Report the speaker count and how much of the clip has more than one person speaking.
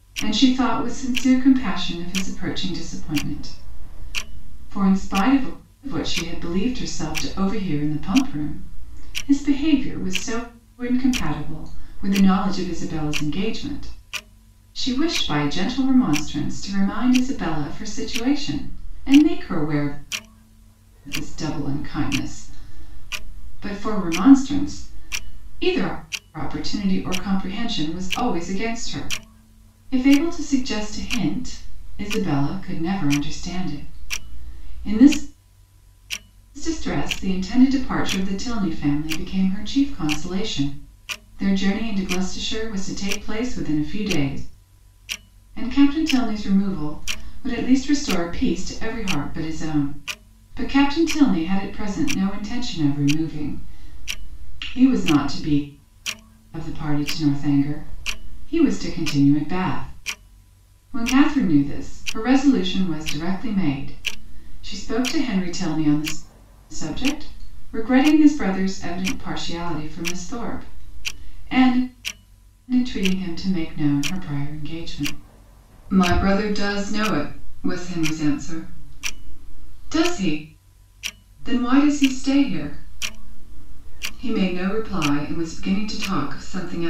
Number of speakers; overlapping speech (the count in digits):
1, no overlap